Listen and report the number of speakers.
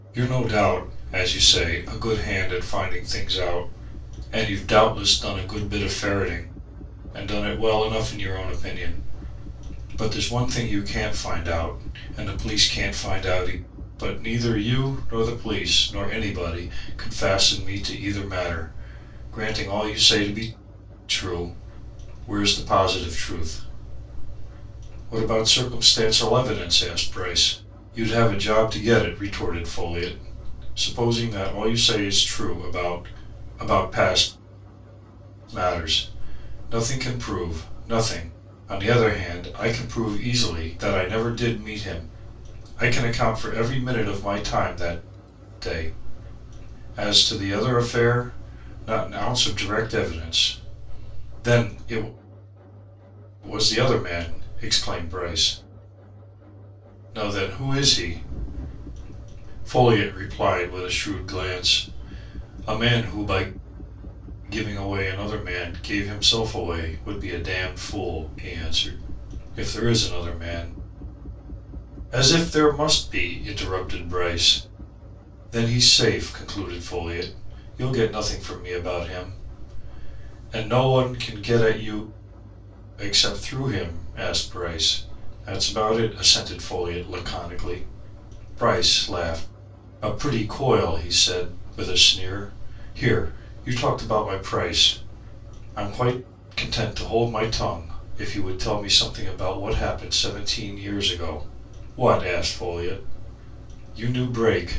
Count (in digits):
1